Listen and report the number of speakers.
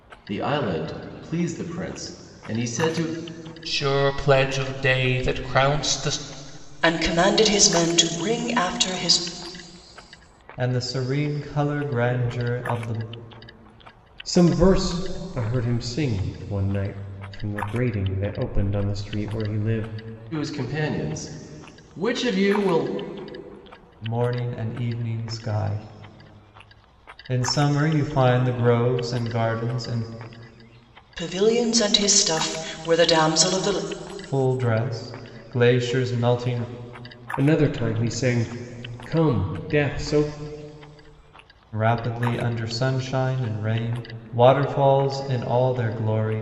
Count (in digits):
5